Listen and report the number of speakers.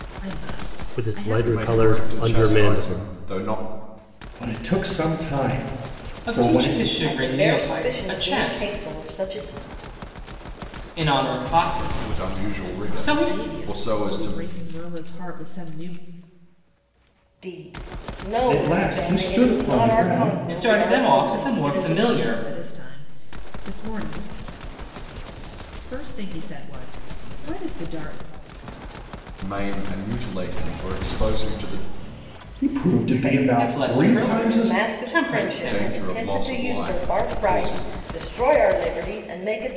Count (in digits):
6